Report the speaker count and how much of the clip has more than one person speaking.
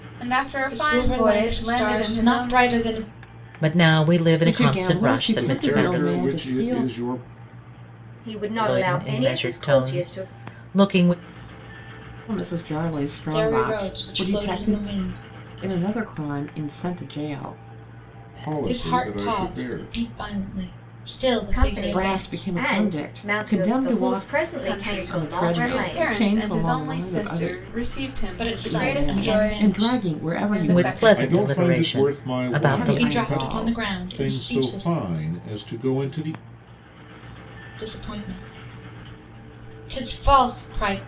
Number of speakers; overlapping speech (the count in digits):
6, about 50%